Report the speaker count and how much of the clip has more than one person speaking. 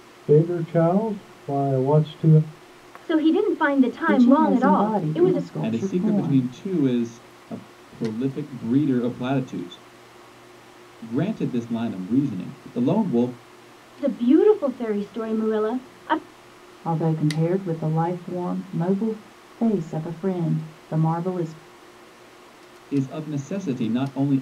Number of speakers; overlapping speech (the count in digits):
4, about 10%